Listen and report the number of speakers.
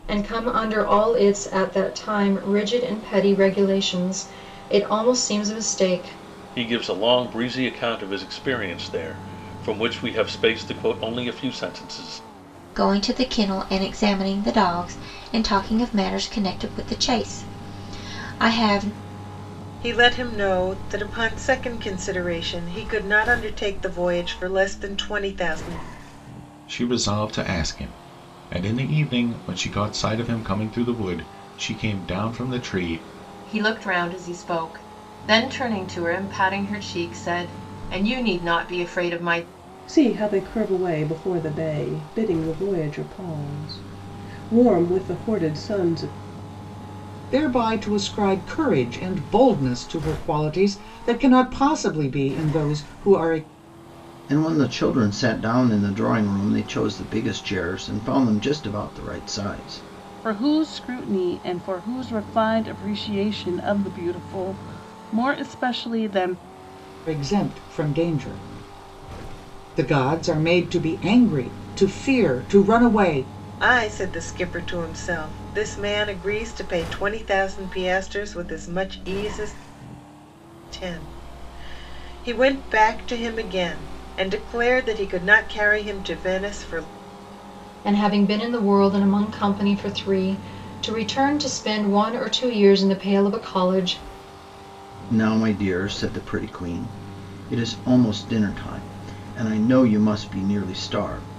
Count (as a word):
ten